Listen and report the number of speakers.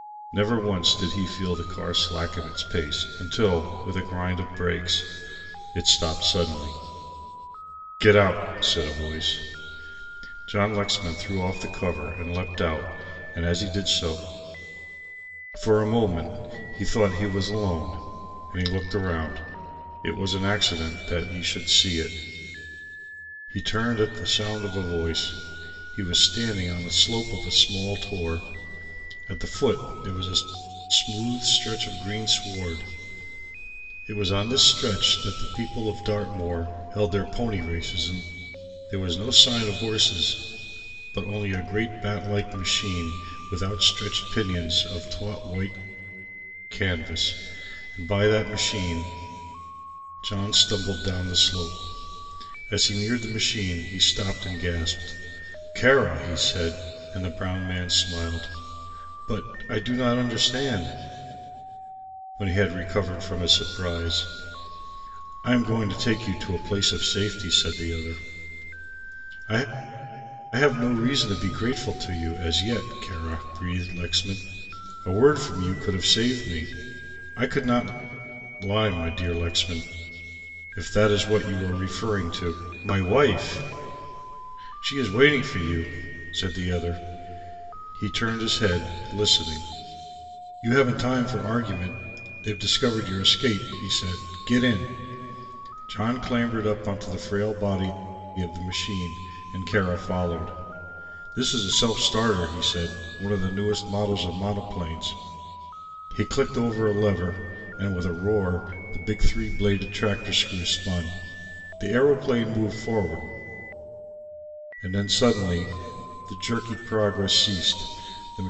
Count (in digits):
1